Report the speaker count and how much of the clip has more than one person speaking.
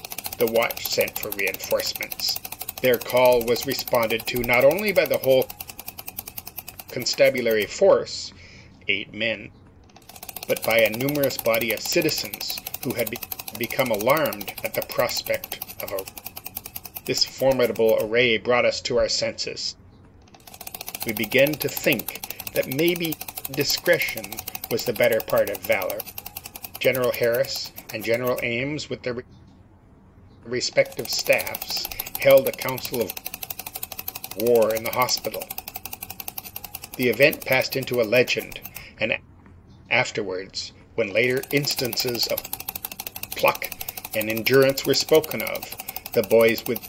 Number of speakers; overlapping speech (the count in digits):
1, no overlap